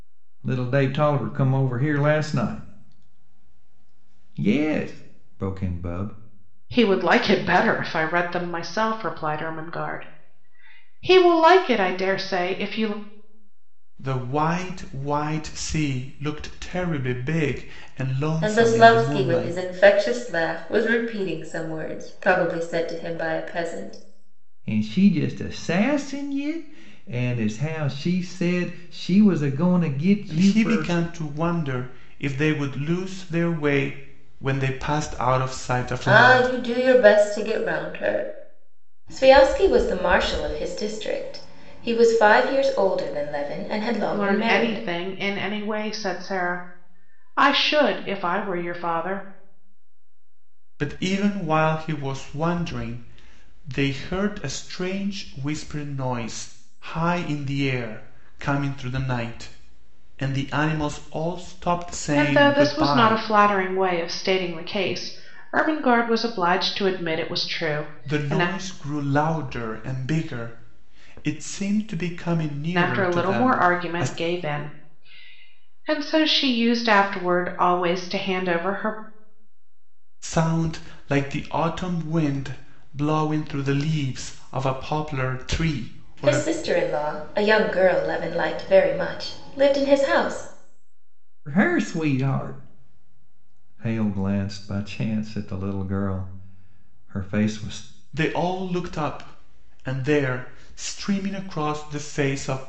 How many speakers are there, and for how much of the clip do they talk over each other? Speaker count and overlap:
four, about 6%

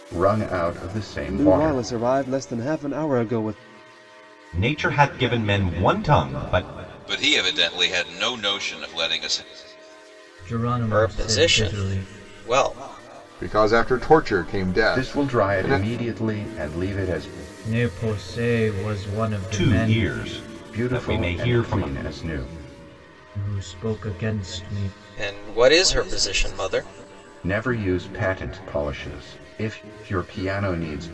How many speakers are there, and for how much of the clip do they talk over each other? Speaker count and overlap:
seven, about 15%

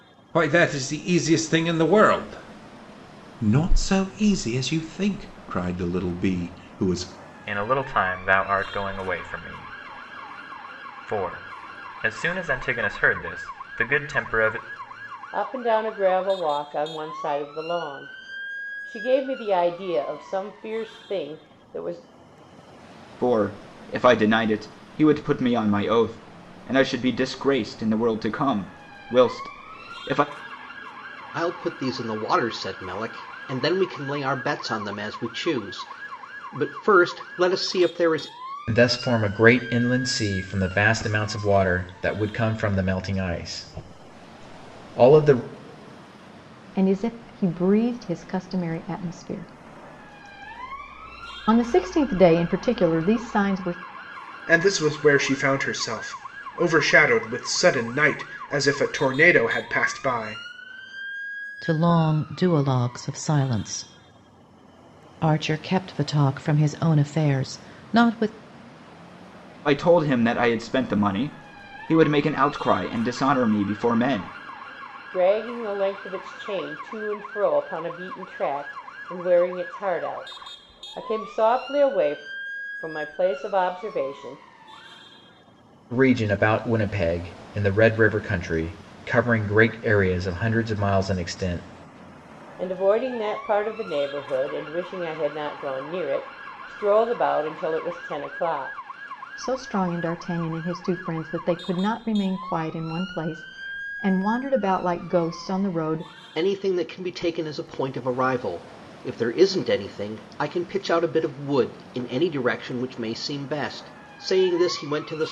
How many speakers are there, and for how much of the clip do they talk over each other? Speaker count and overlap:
nine, no overlap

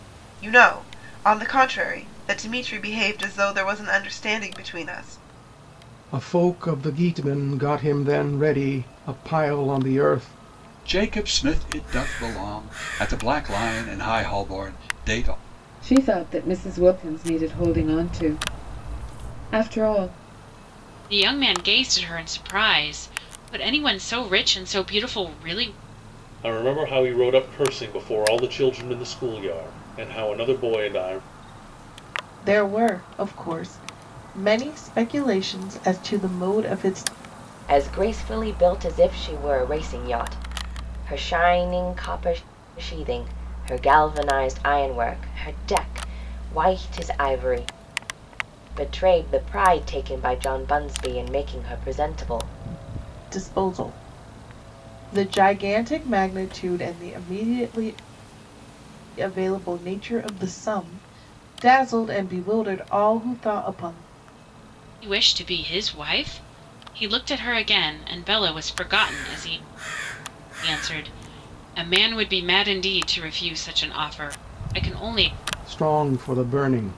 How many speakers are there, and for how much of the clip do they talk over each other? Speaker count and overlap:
eight, no overlap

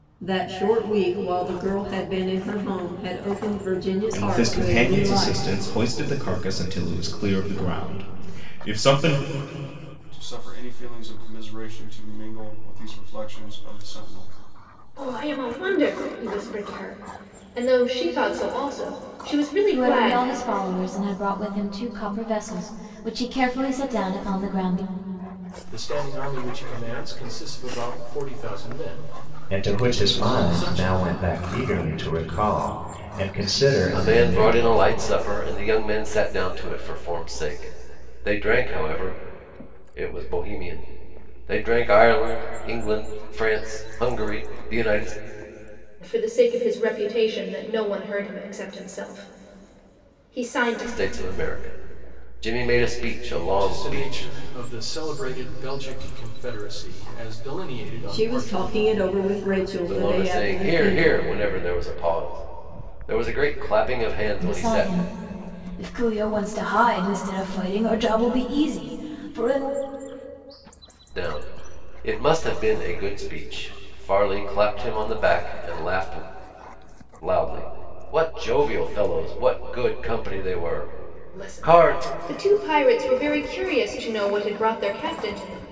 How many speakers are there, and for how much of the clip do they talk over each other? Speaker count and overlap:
eight, about 10%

